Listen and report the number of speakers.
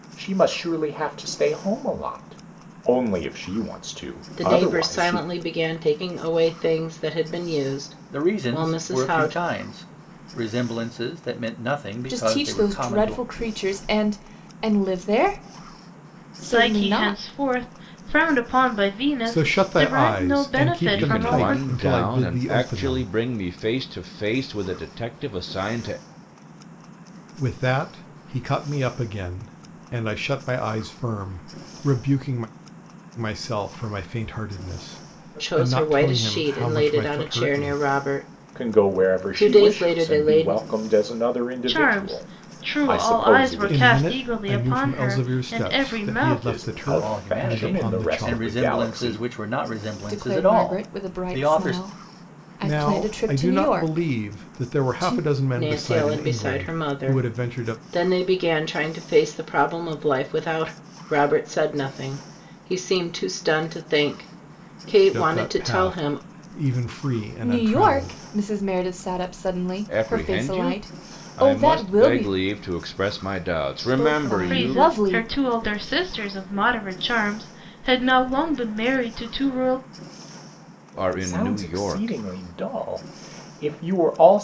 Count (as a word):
seven